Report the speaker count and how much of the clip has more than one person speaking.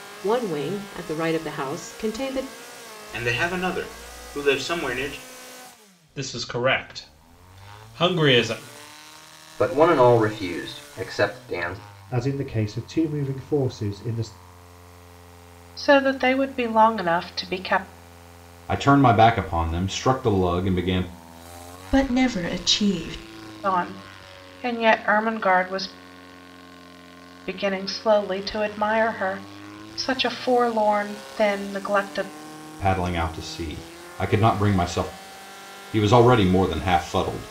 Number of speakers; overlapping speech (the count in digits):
8, no overlap